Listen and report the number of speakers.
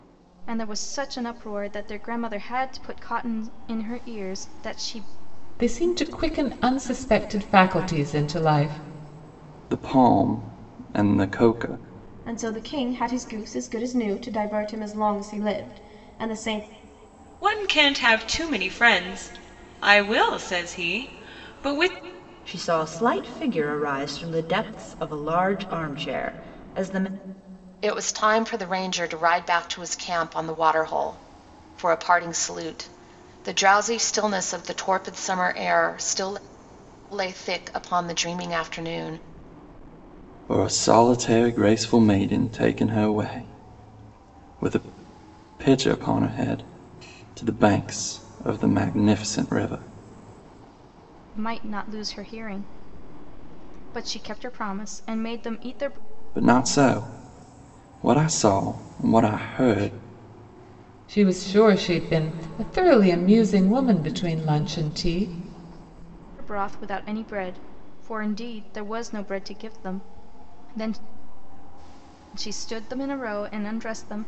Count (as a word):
seven